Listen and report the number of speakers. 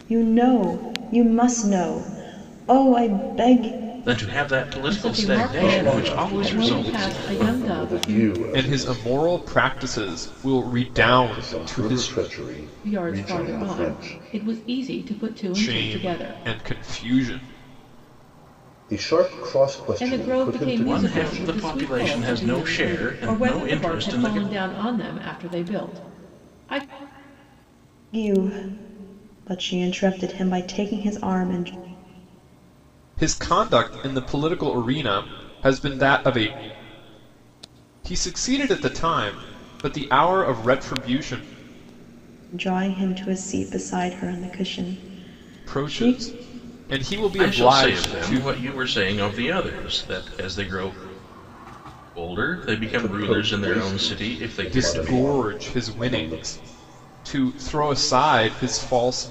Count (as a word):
five